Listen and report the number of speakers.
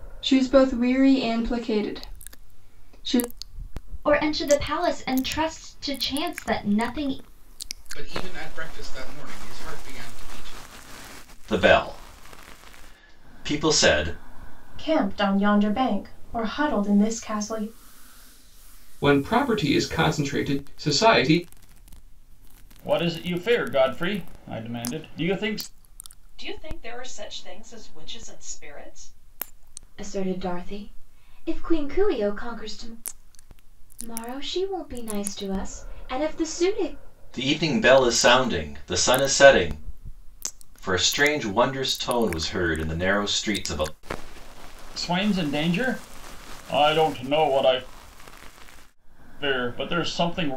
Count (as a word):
nine